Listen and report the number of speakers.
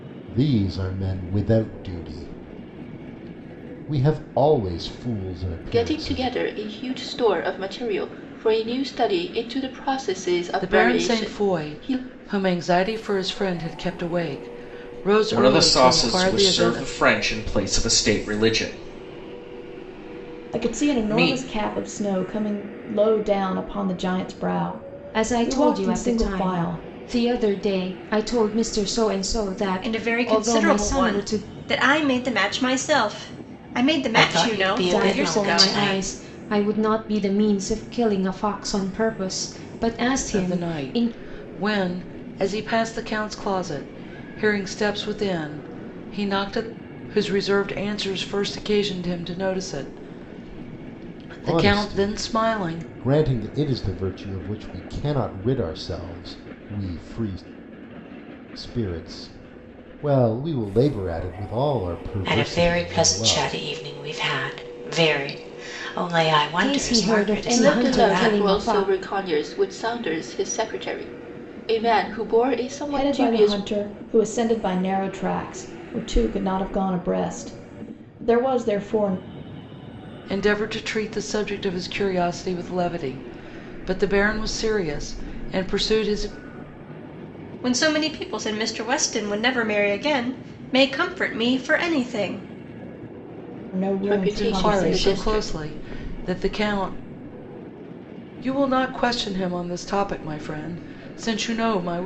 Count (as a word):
eight